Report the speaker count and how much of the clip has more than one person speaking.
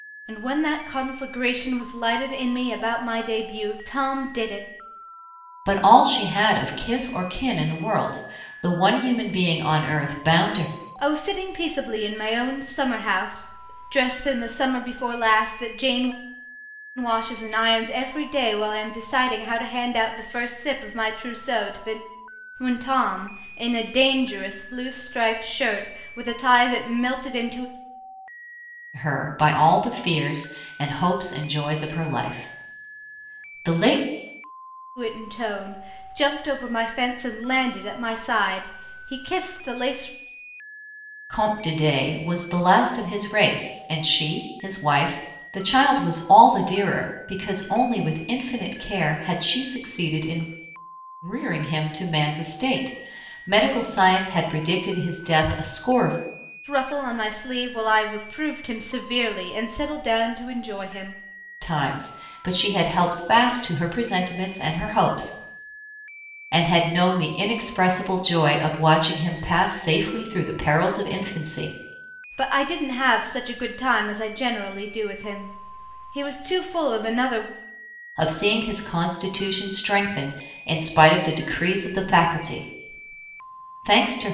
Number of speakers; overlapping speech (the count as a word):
two, no overlap